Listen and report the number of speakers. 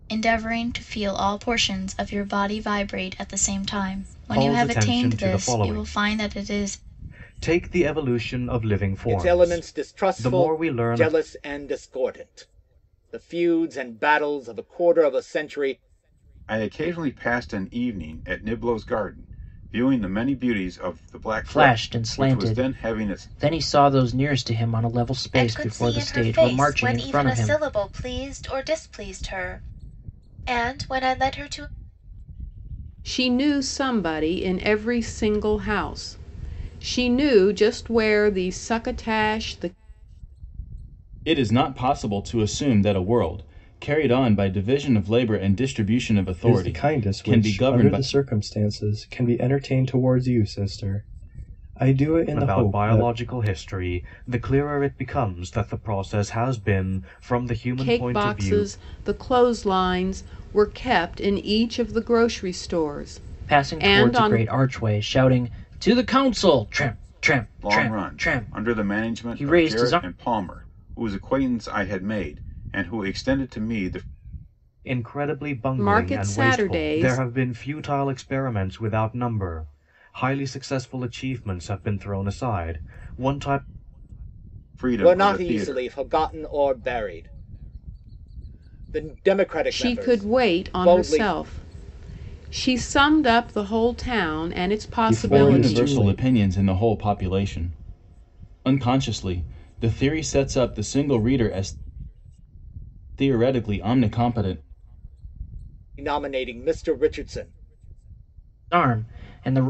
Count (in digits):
9